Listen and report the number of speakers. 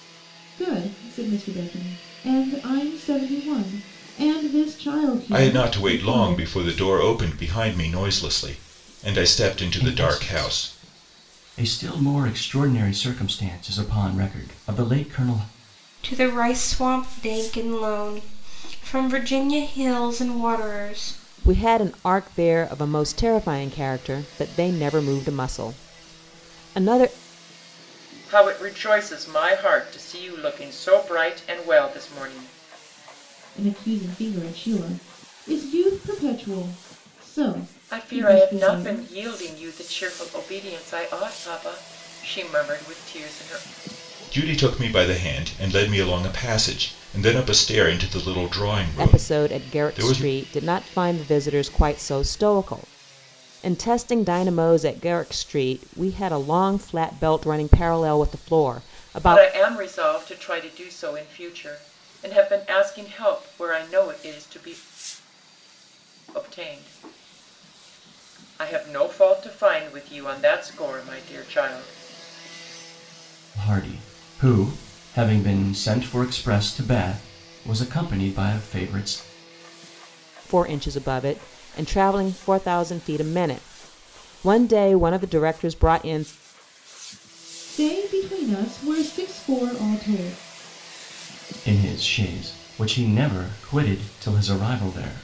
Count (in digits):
6